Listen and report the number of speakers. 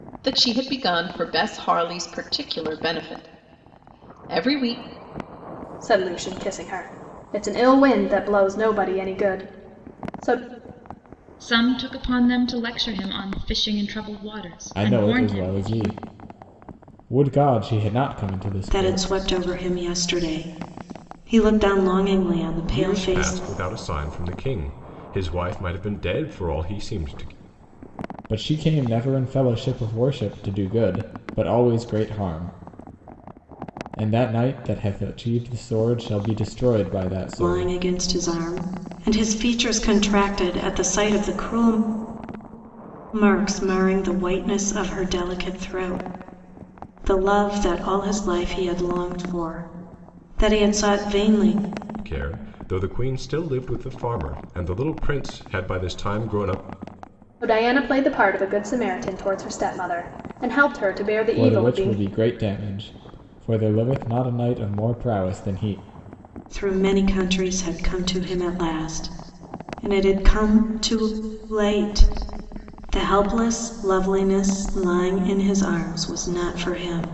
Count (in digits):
6